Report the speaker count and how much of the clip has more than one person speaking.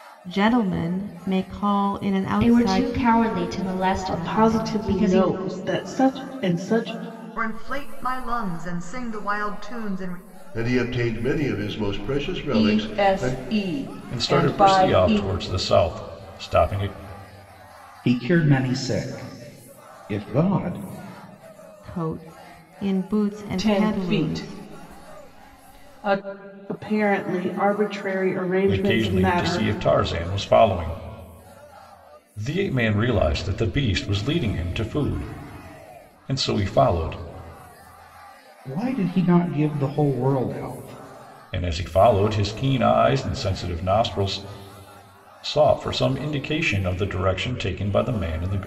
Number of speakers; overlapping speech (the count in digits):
8, about 12%